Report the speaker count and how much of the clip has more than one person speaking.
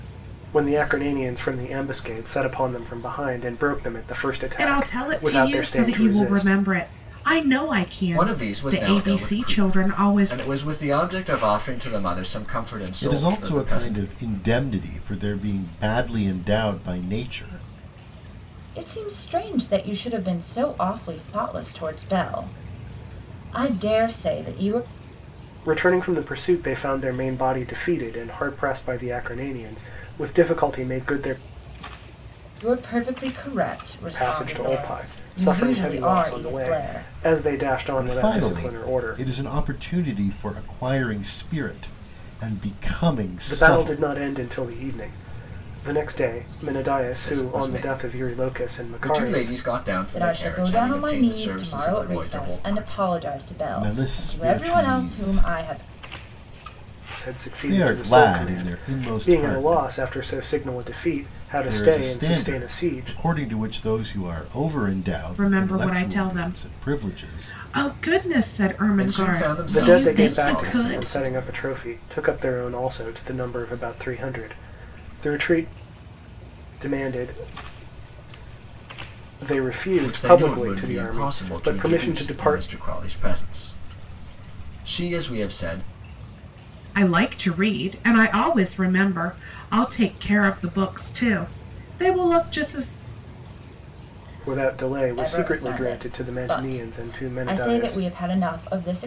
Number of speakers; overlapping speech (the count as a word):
five, about 33%